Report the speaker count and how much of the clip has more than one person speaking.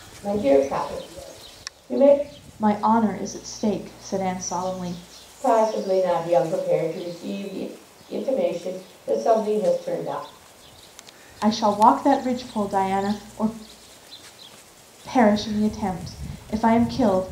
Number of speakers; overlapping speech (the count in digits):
2, no overlap